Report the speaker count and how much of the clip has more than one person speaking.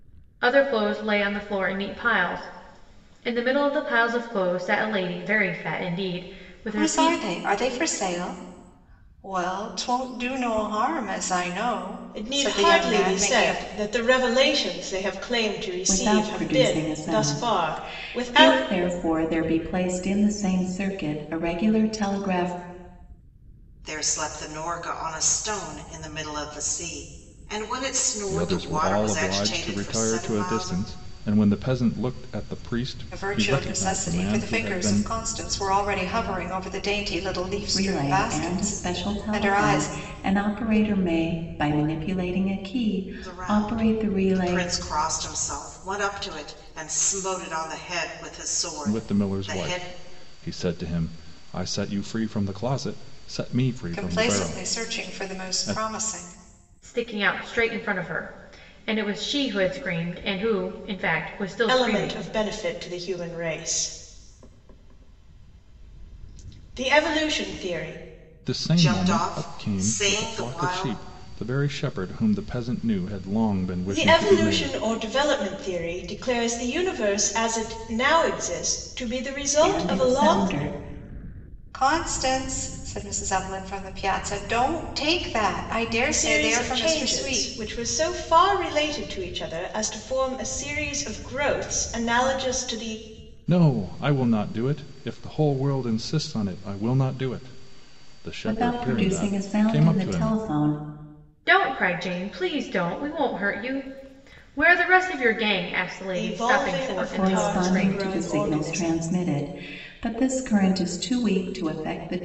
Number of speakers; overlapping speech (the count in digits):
6, about 24%